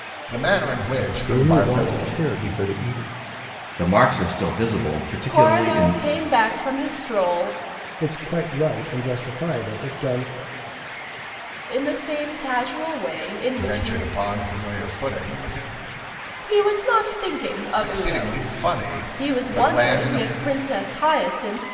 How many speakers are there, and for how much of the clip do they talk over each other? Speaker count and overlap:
5, about 20%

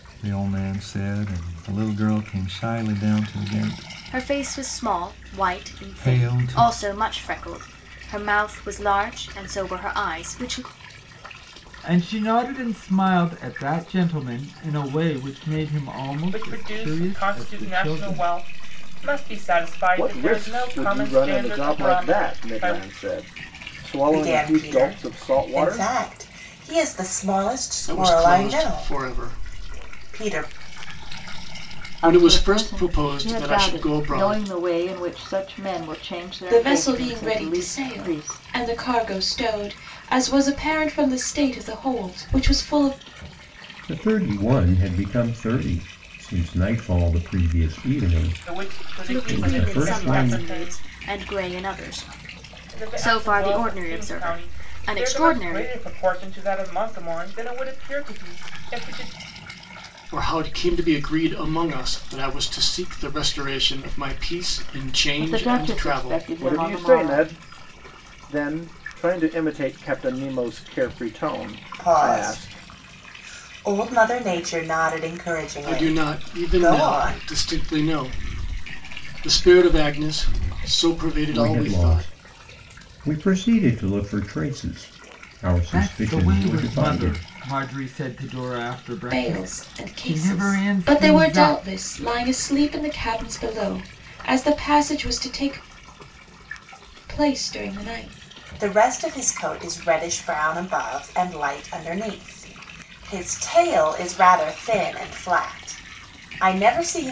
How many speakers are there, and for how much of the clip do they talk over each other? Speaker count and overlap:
10, about 30%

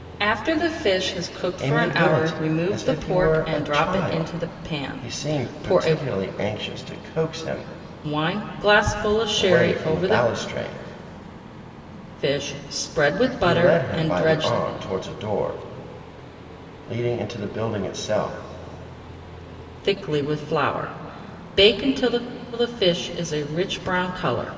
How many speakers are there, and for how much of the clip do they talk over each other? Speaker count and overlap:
2, about 27%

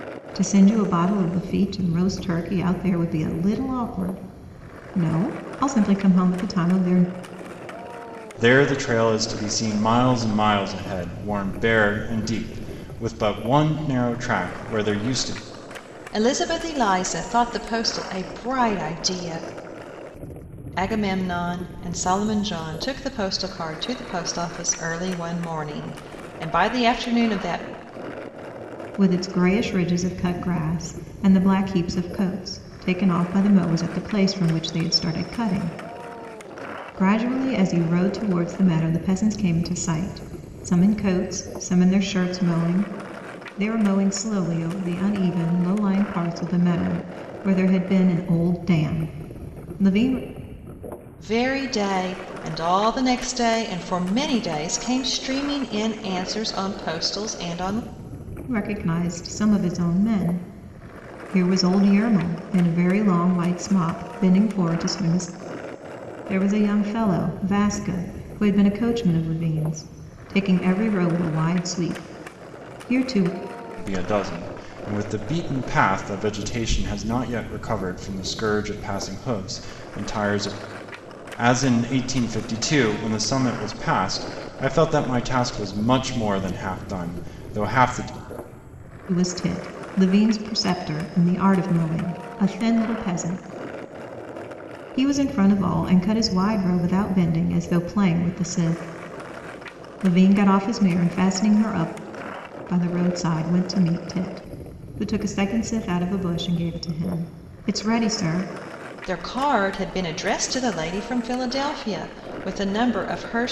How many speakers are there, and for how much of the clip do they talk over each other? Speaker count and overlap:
3, no overlap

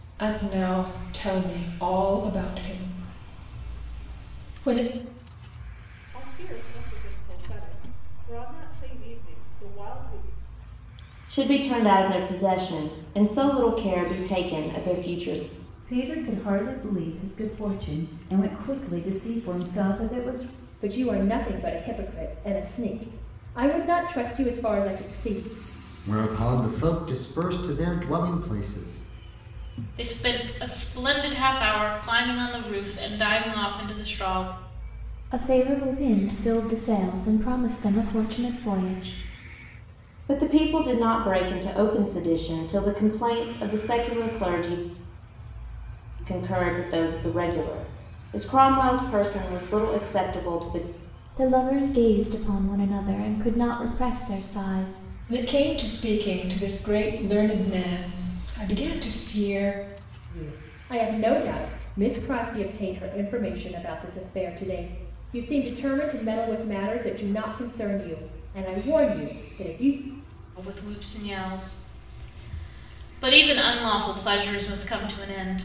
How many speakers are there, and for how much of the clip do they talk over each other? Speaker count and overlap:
8, no overlap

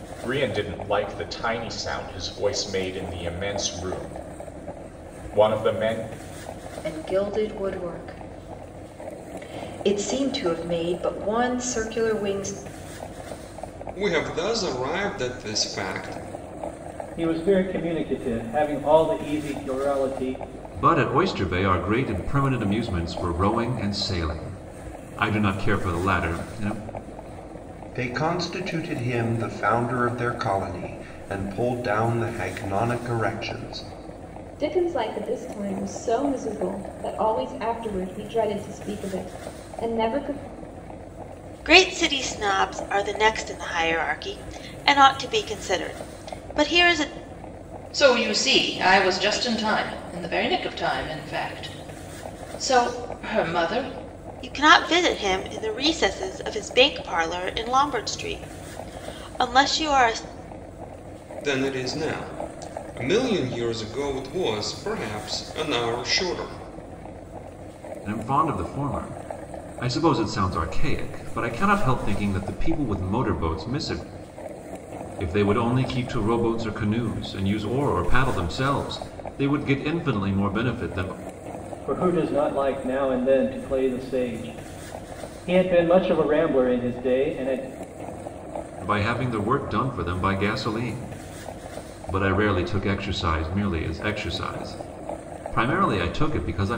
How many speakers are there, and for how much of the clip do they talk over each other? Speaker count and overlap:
9, no overlap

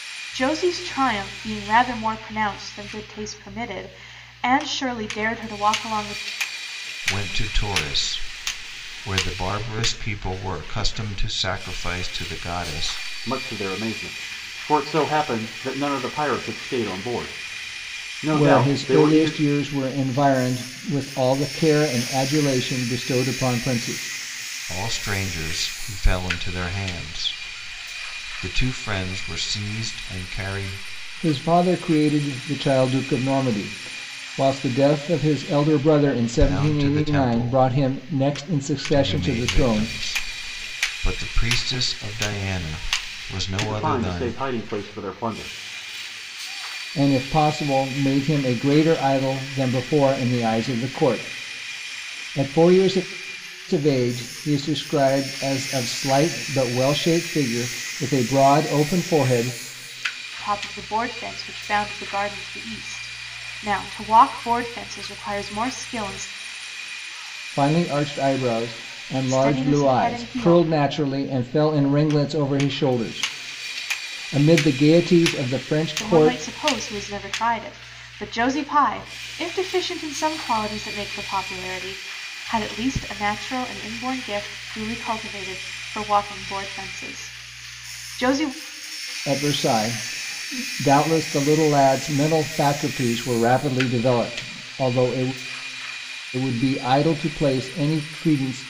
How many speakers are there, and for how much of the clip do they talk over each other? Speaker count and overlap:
4, about 6%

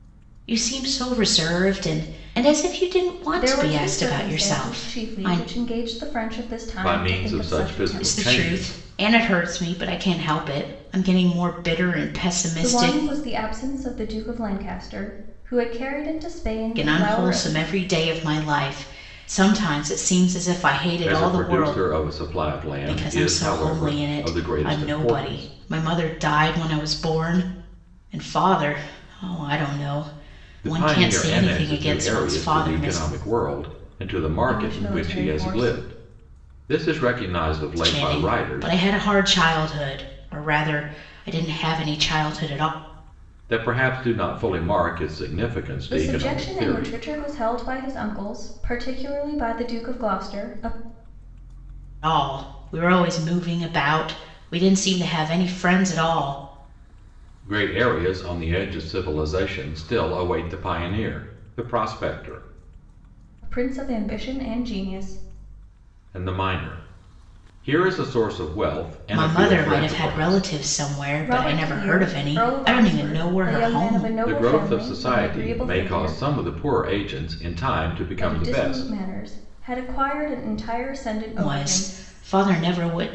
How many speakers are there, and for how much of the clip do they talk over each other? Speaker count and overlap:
3, about 27%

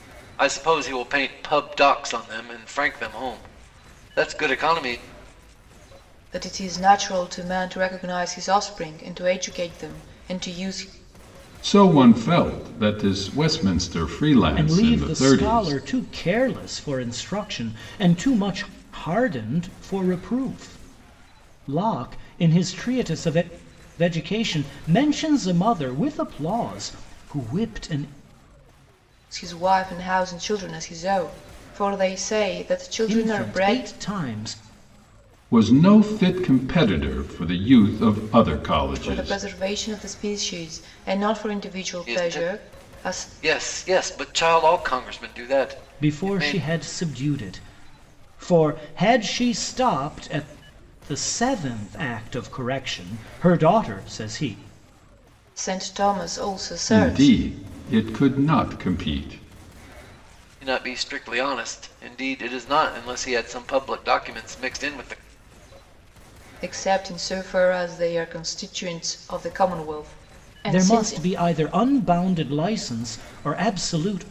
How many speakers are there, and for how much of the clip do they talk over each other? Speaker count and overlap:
4, about 7%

